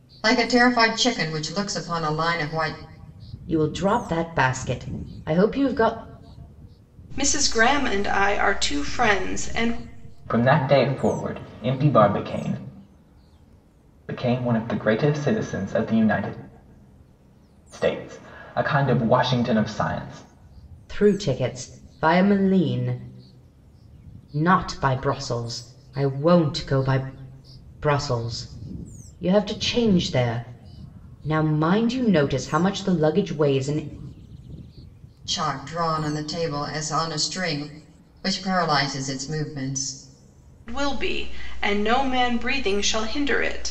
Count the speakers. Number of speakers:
four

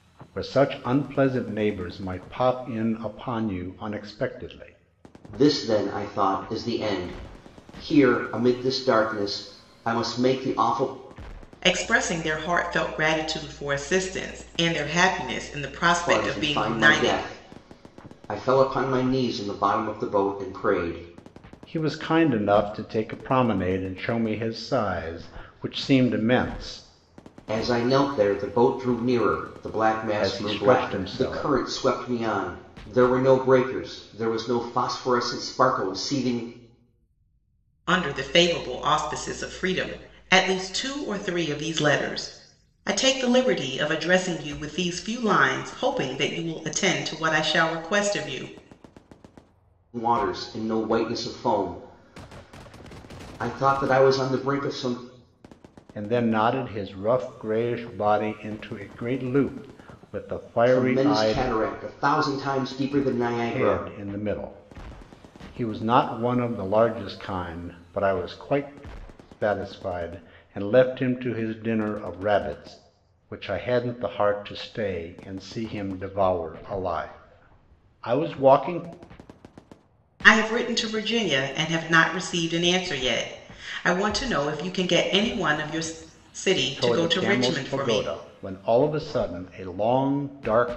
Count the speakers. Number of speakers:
three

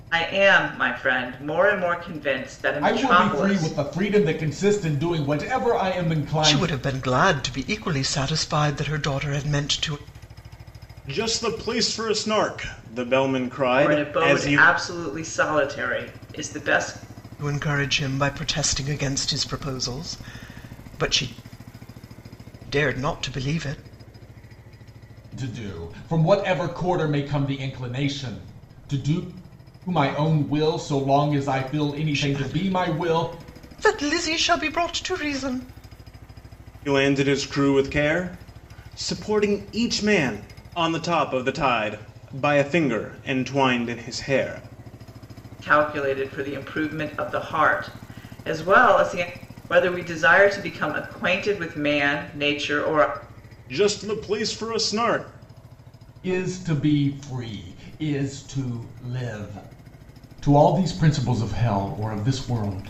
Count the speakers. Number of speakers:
four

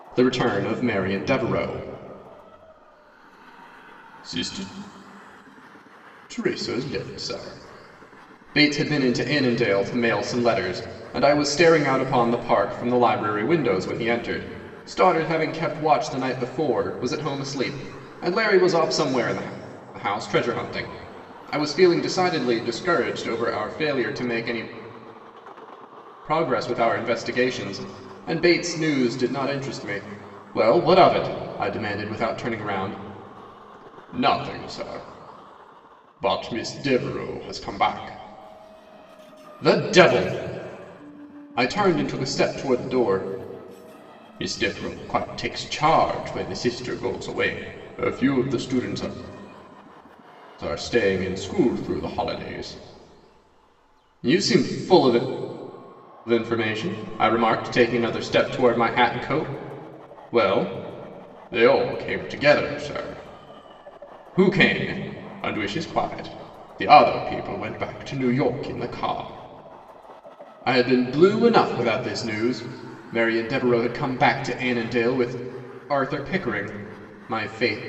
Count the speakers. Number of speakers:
one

